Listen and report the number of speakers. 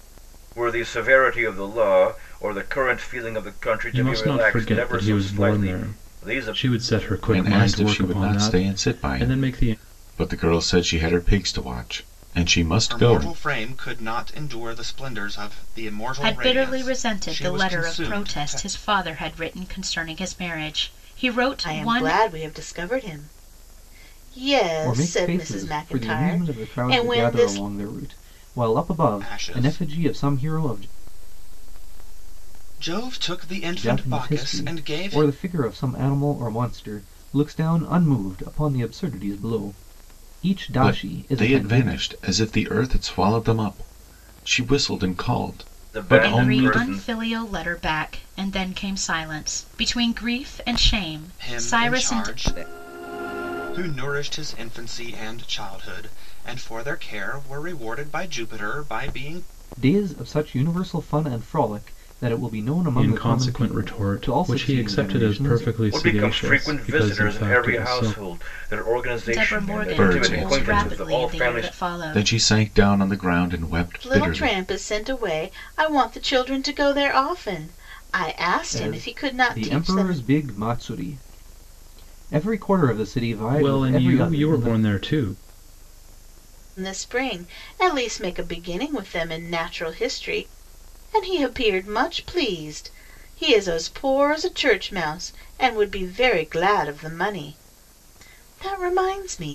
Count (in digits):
7